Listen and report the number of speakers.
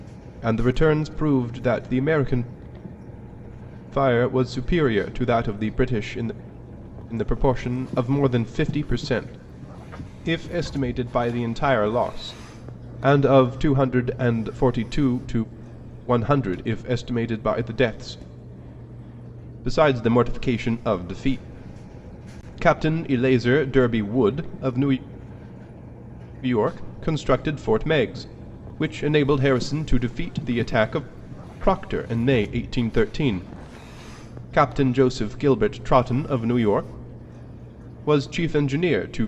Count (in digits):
1